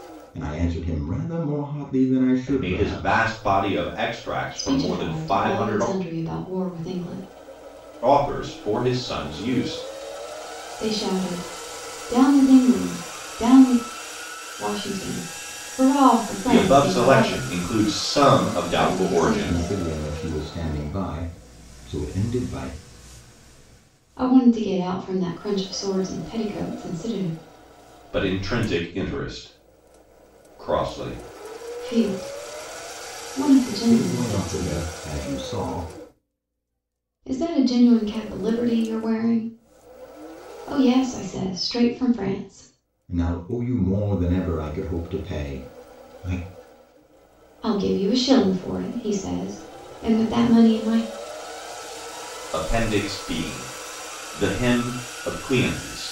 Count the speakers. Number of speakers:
3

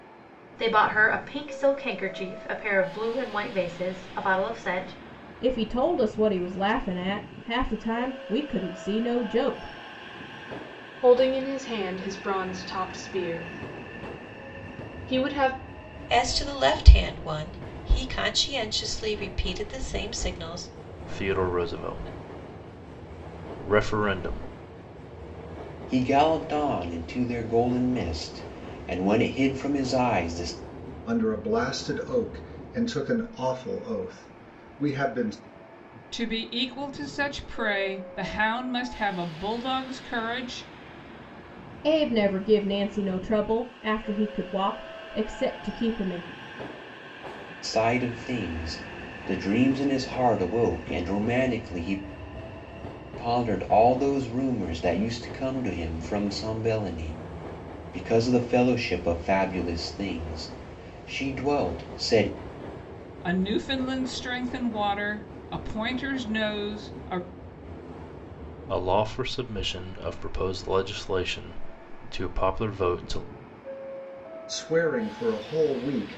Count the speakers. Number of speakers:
8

